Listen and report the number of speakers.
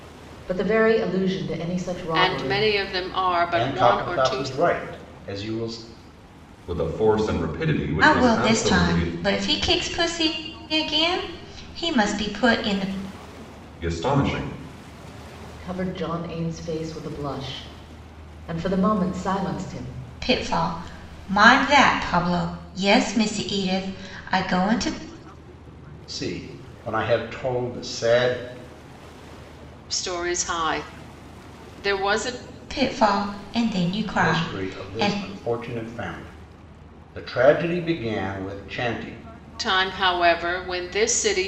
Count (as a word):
five